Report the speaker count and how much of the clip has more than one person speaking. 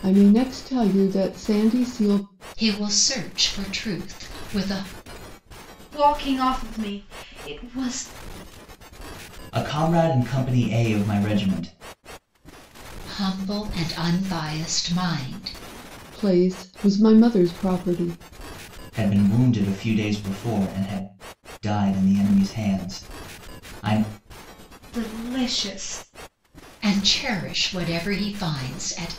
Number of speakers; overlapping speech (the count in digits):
4, no overlap